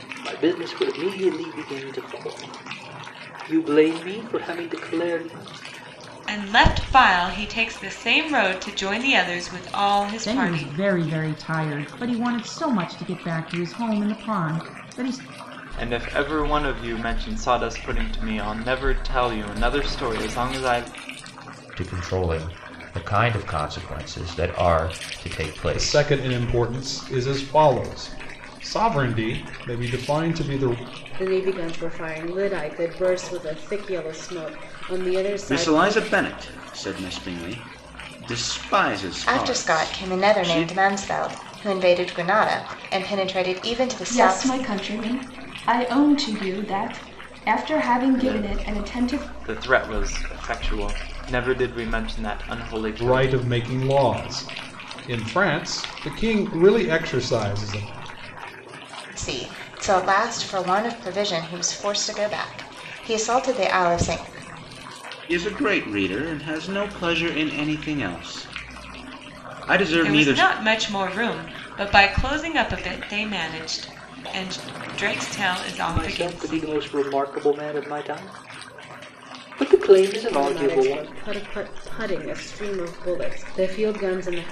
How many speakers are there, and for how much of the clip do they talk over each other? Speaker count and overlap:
10, about 9%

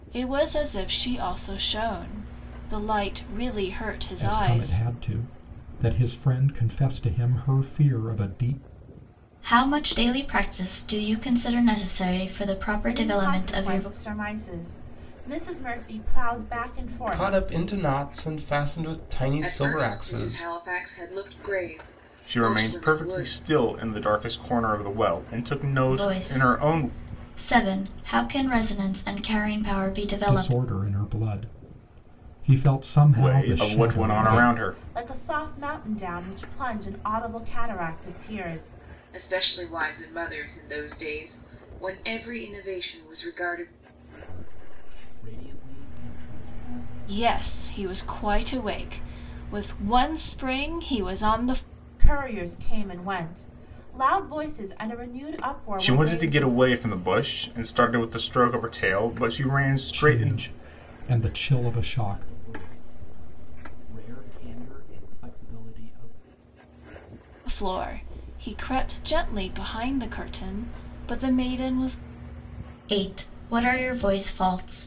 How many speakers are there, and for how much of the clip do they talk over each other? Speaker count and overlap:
8, about 16%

